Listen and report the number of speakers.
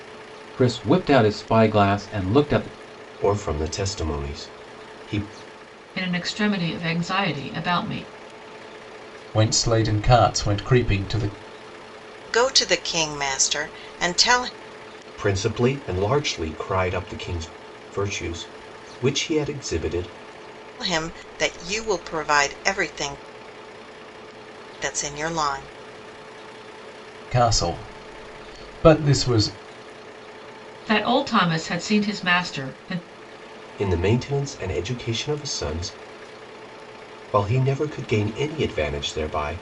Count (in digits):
5